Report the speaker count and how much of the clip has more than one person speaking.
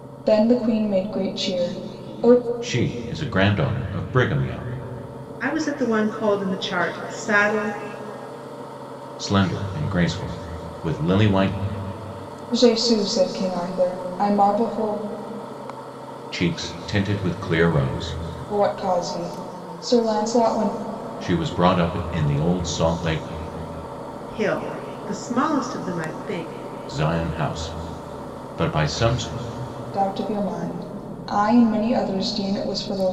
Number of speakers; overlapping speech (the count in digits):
3, no overlap